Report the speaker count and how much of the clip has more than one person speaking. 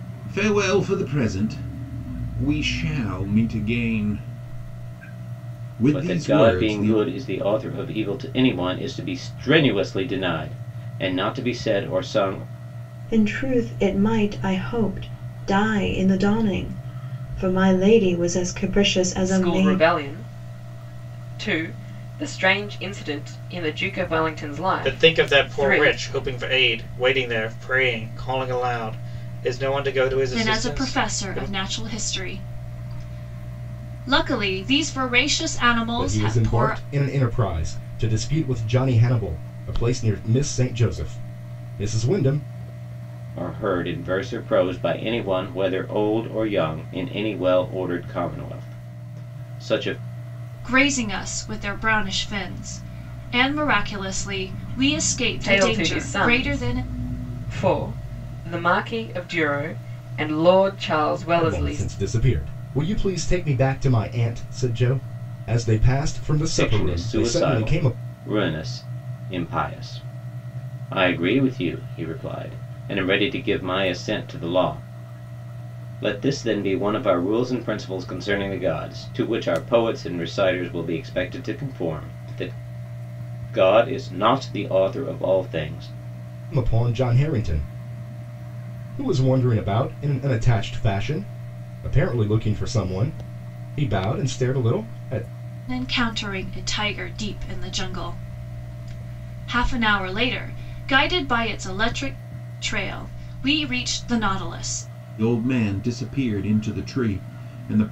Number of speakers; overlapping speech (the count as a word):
seven, about 8%